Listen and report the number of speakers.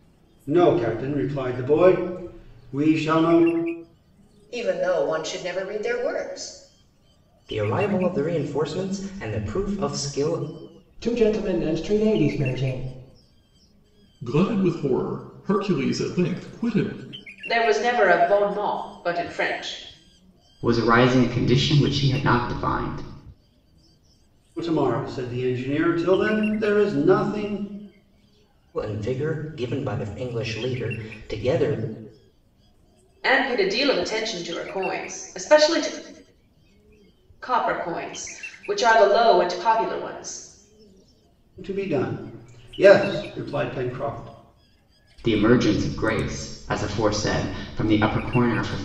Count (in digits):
7